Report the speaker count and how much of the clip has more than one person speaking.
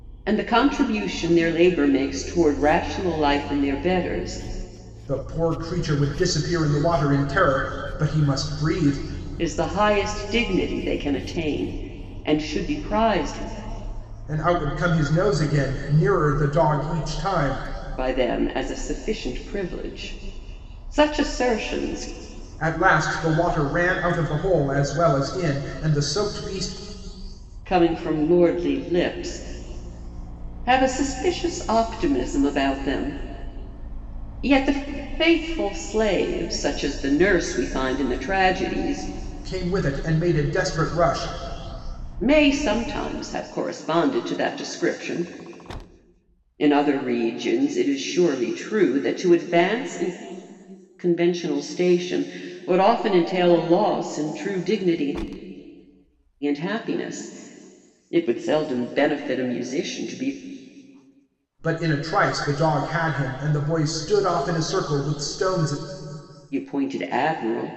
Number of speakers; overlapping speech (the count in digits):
2, no overlap